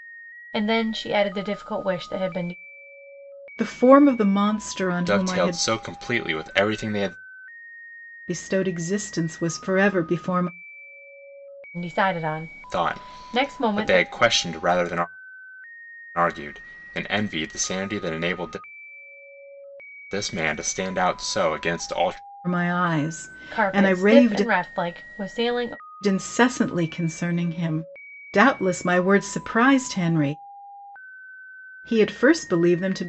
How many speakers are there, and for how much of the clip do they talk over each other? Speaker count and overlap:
3, about 10%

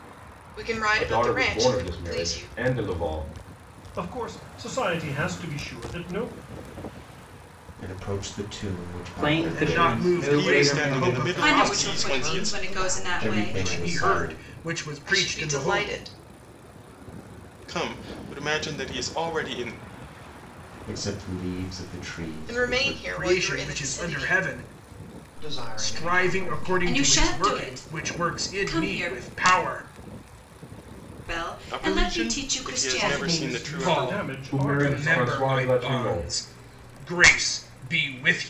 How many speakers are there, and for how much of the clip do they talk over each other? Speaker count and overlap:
9, about 47%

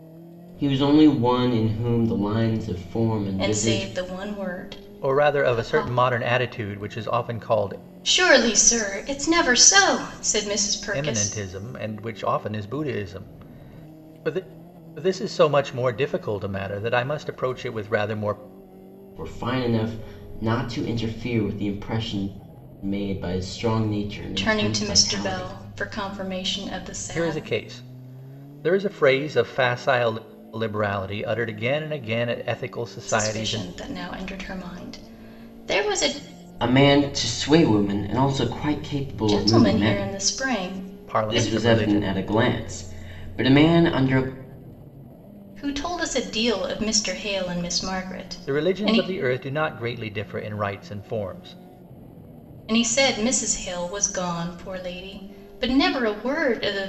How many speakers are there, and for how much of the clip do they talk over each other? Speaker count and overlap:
3, about 12%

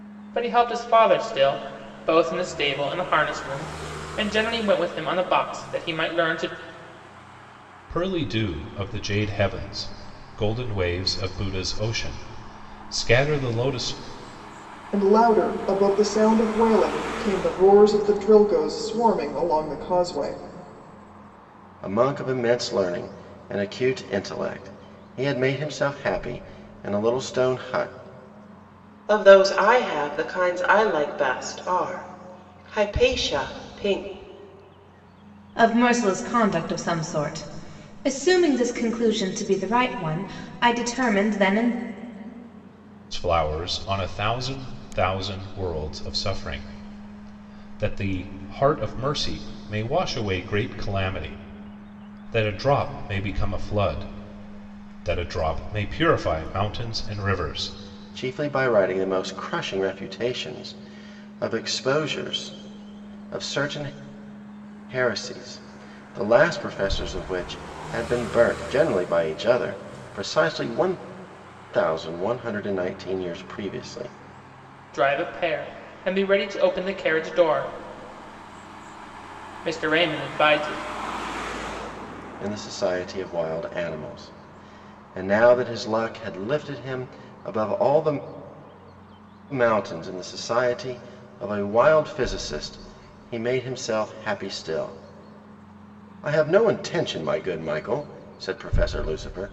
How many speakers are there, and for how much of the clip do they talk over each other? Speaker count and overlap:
6, no overlap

